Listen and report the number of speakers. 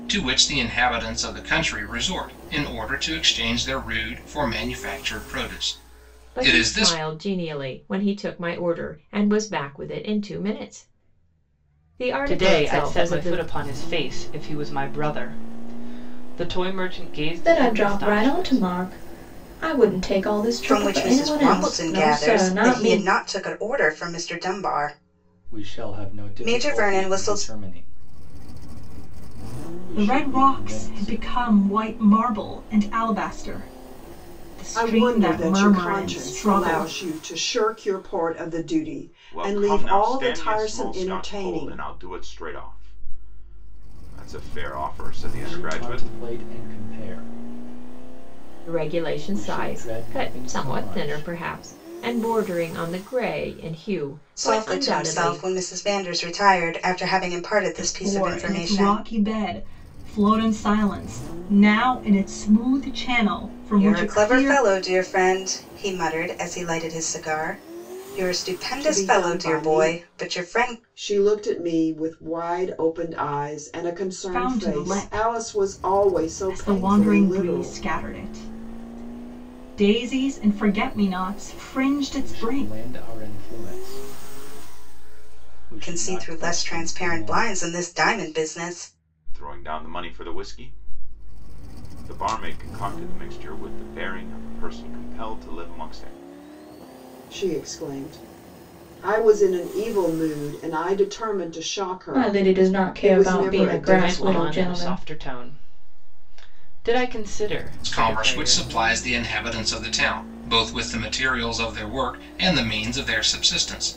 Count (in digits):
9